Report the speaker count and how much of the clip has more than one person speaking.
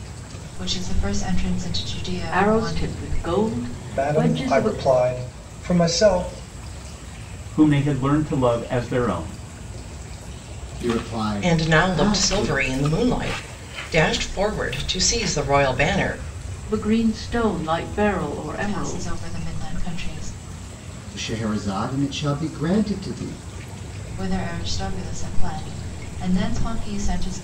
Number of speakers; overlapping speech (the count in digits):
6, about 11%